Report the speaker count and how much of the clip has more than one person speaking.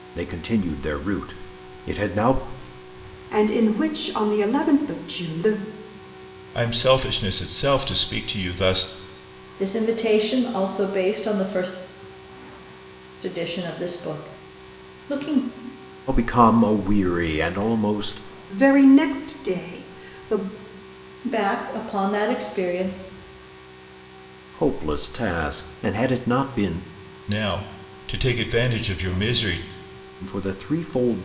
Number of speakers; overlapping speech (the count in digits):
4, no overlap